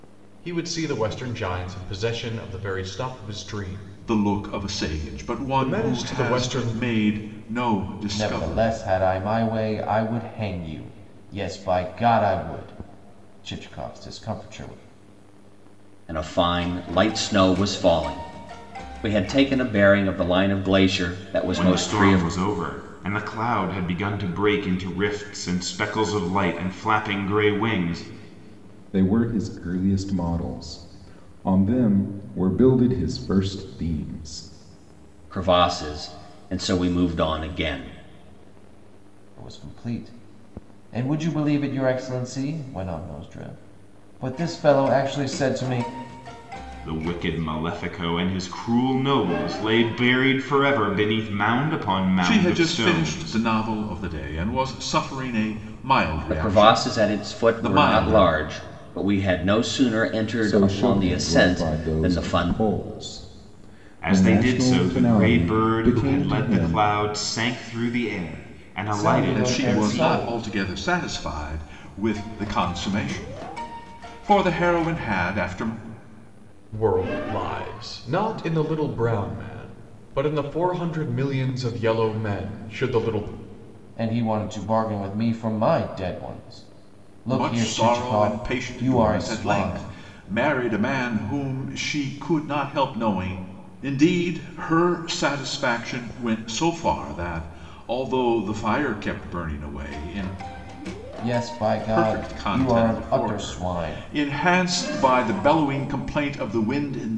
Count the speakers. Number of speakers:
six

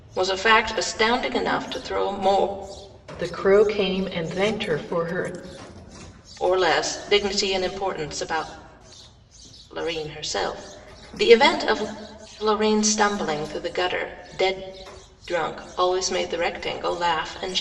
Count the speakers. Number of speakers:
two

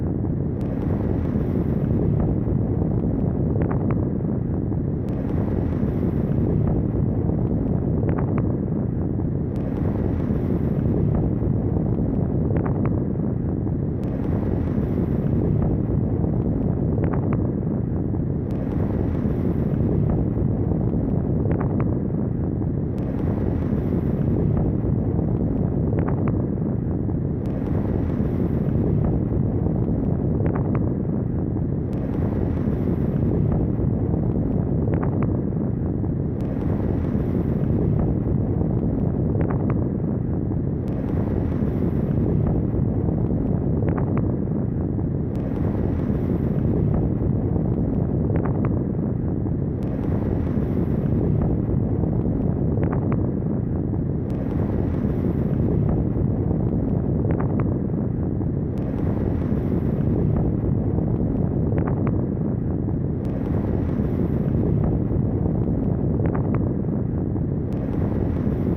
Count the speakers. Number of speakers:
zero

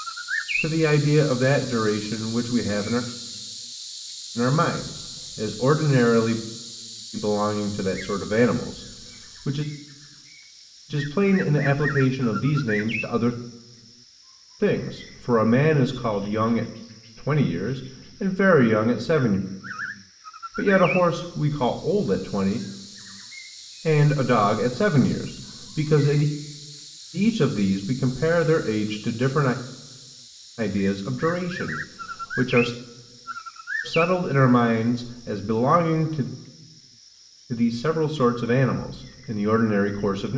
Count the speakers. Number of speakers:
one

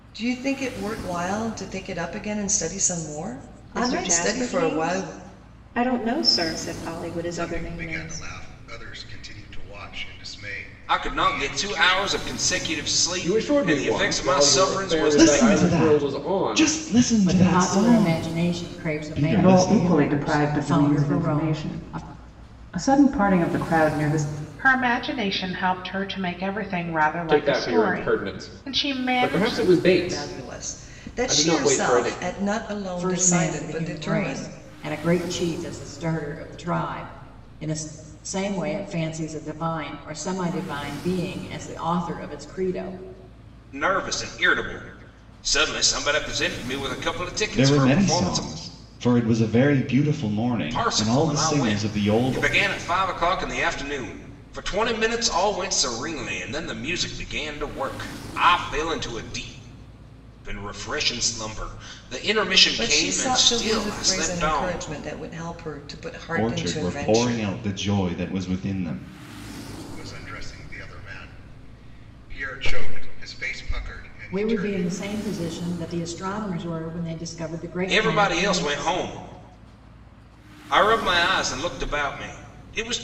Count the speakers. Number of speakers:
nine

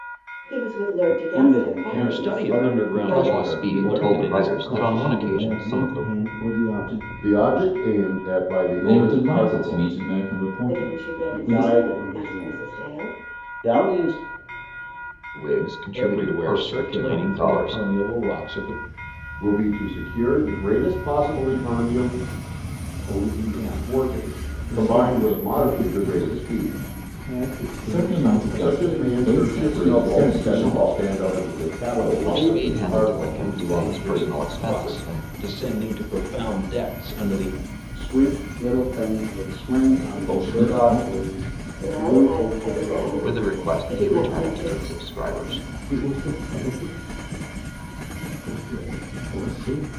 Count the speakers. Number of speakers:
seven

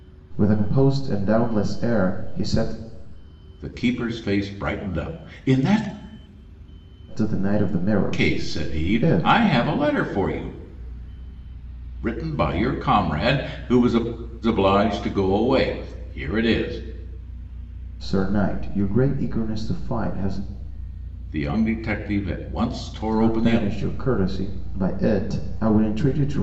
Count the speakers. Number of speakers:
two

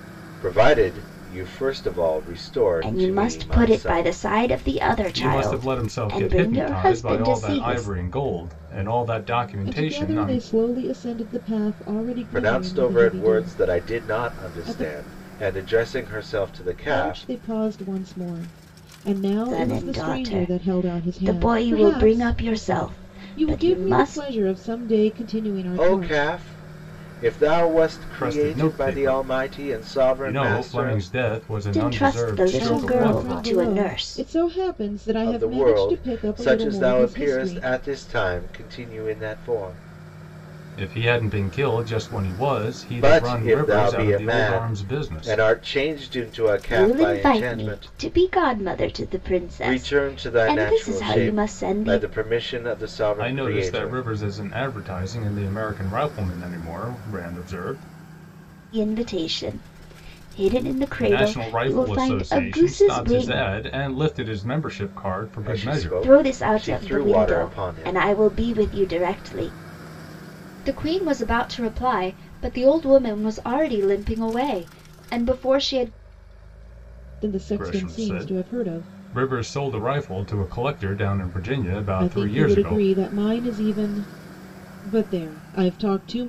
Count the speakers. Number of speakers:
four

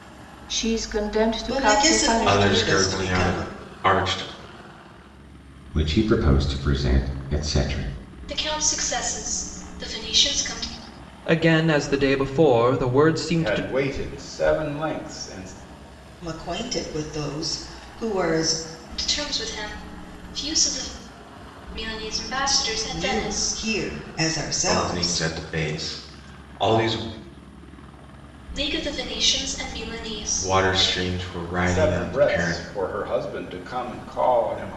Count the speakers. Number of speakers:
seven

